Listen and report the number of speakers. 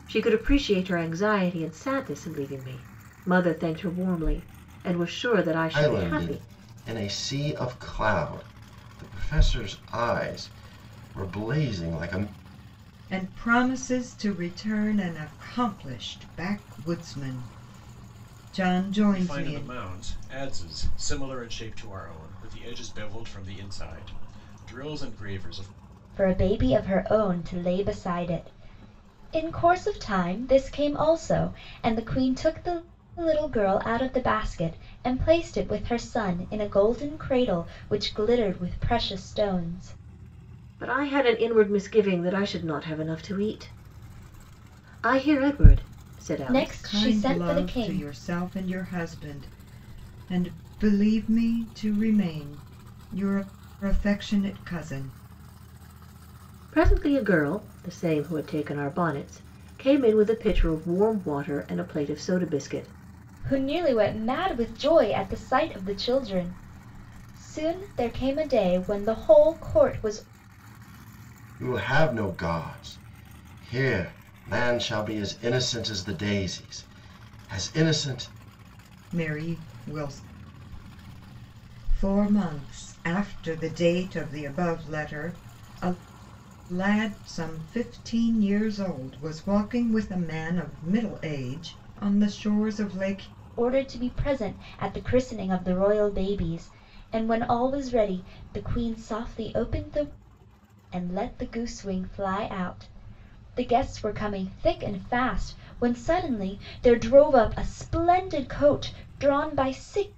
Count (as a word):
five